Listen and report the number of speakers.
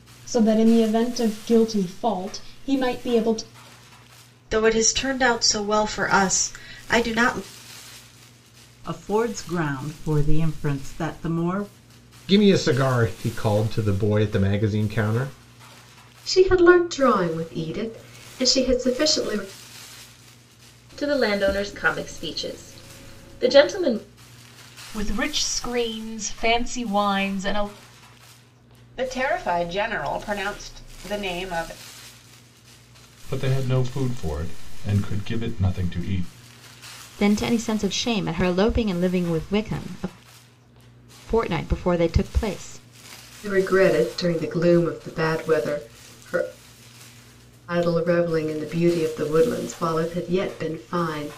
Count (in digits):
10